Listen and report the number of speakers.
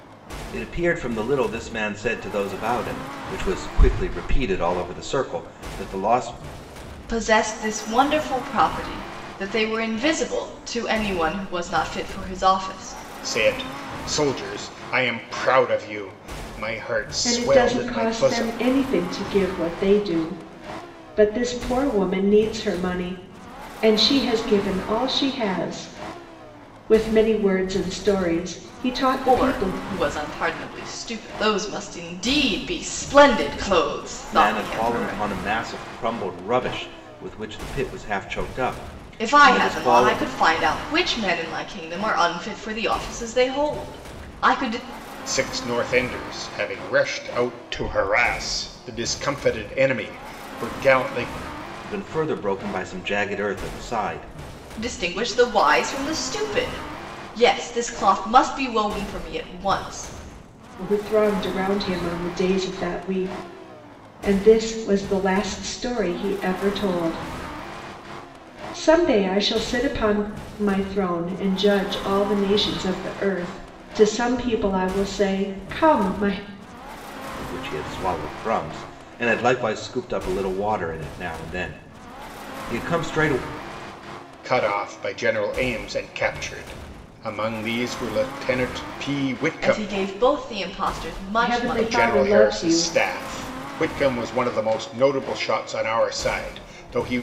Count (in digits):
4